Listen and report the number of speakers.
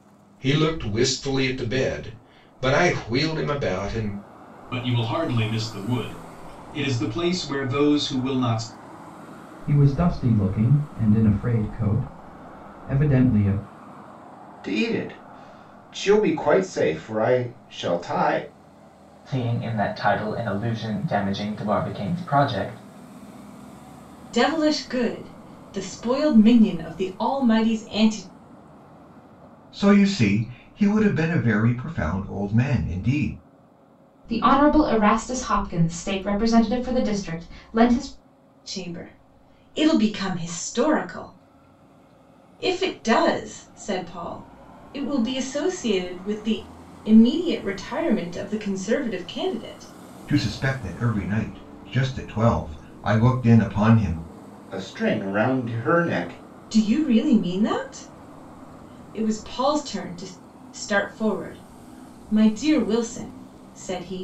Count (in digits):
8